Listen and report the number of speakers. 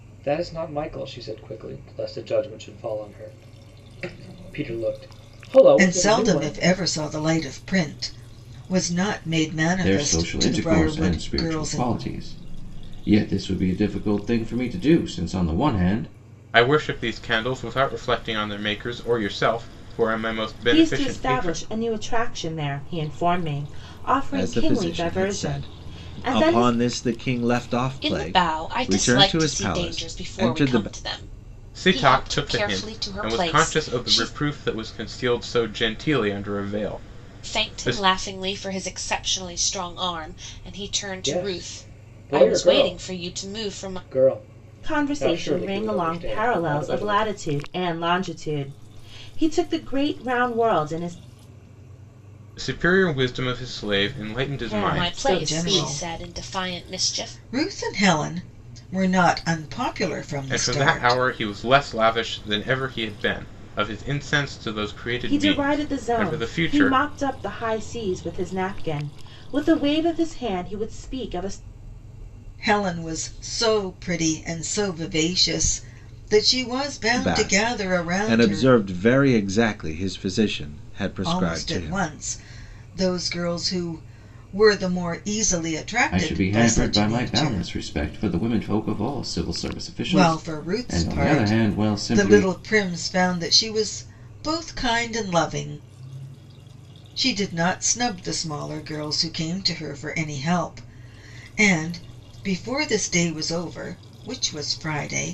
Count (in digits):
7